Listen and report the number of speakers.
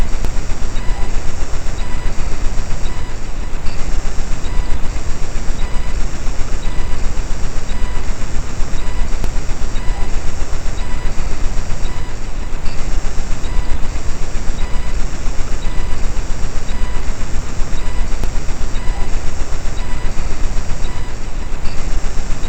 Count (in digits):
0